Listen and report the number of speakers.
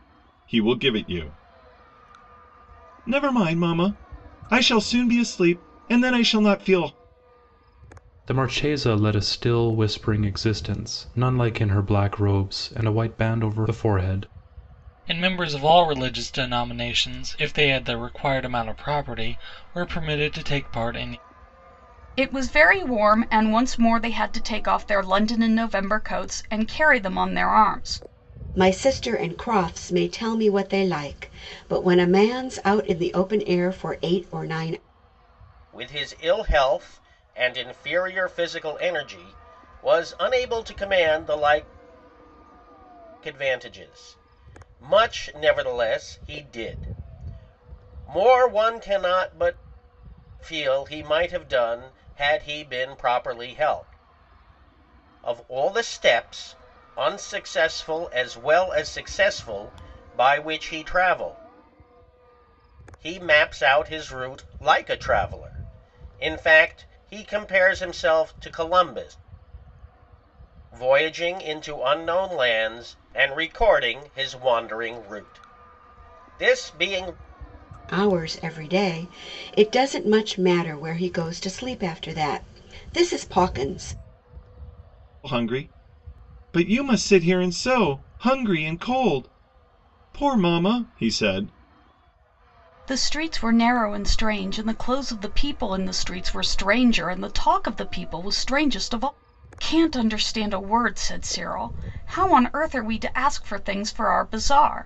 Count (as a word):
six